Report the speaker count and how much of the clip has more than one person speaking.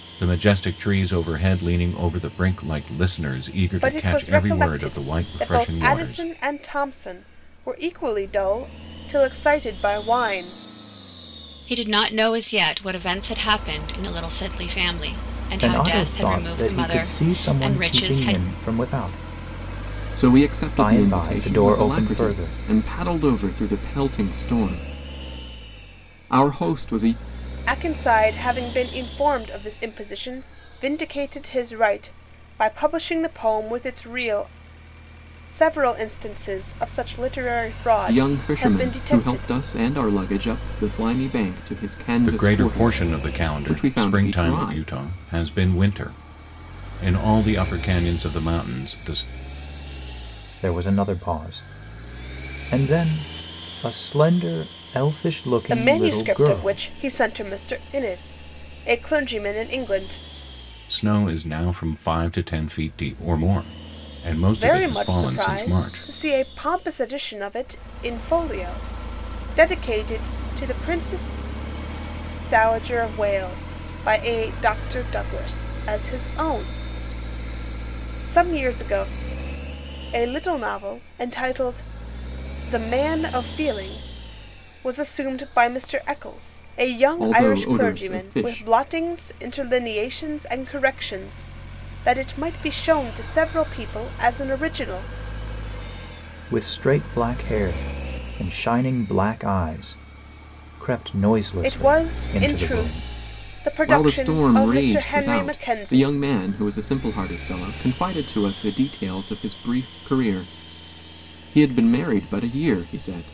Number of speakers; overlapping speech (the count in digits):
5, about 18%